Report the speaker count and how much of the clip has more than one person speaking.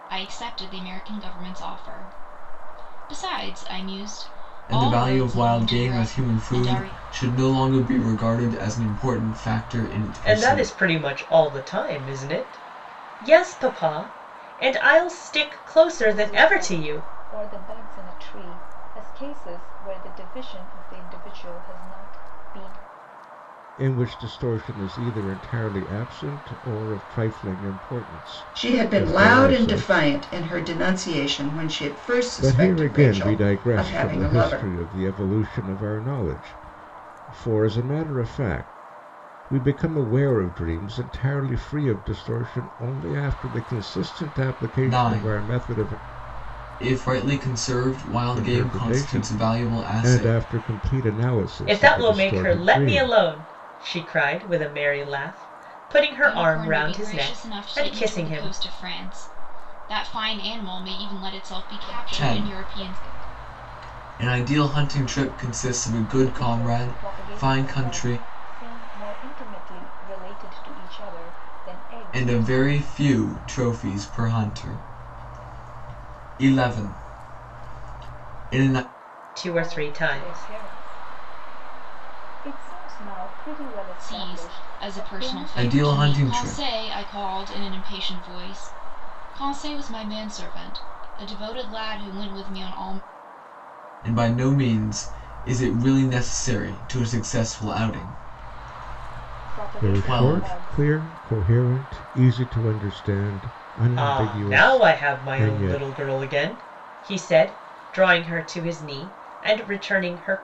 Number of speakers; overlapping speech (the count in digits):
6, about 24%